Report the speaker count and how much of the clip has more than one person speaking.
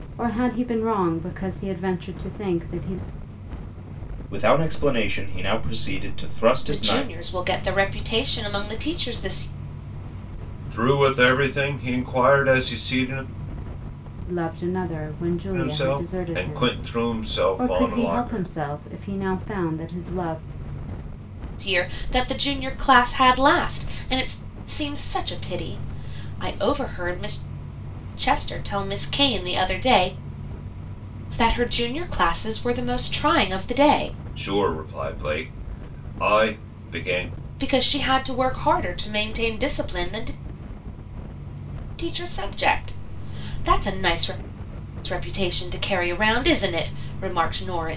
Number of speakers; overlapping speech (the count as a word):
four, about 6%